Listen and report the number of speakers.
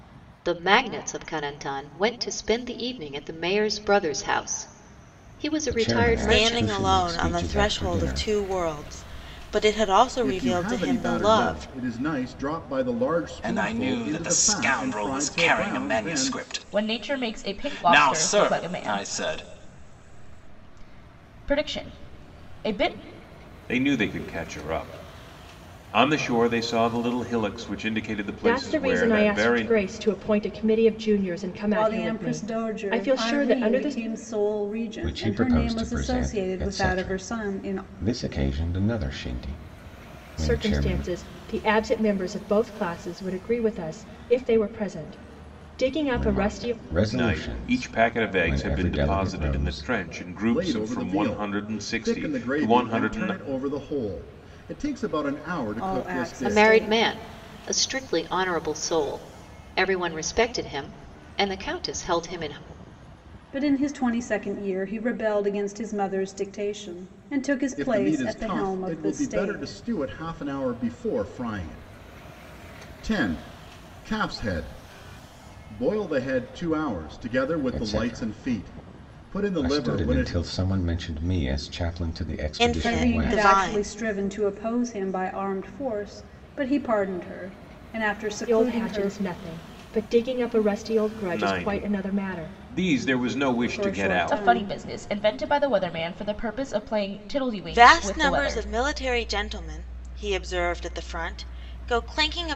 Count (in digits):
9